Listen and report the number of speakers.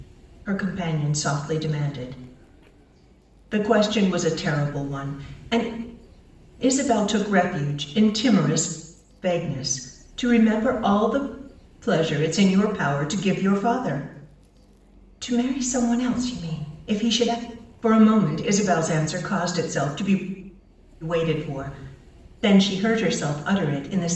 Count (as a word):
one